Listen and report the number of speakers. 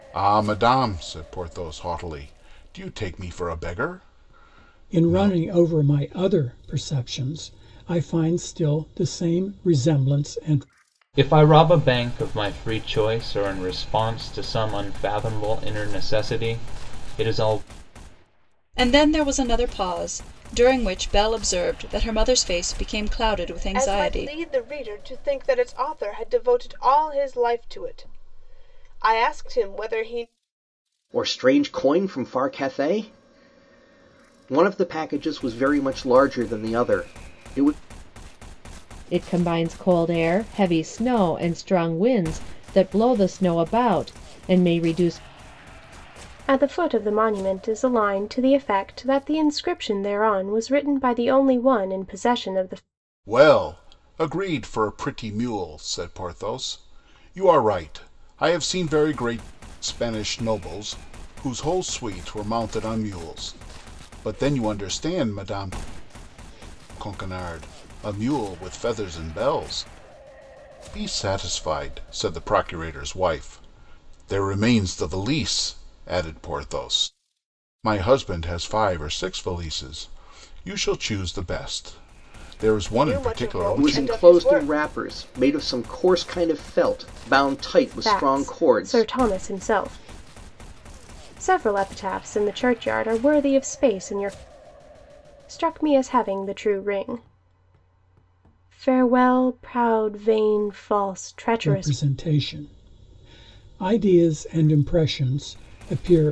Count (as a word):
eight